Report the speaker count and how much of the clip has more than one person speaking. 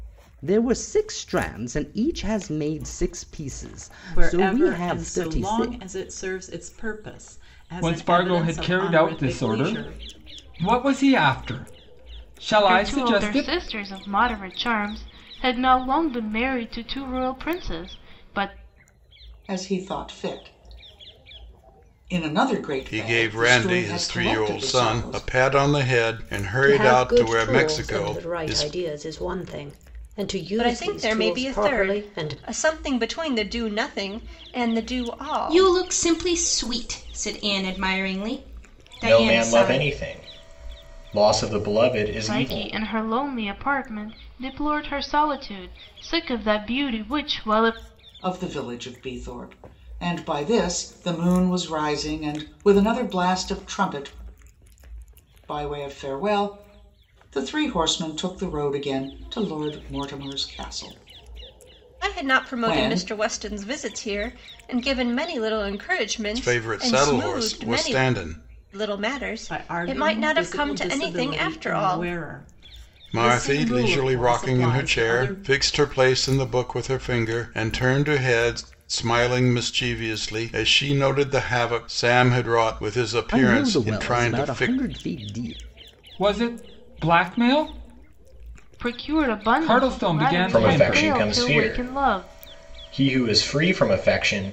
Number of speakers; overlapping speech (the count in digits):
10, about 29%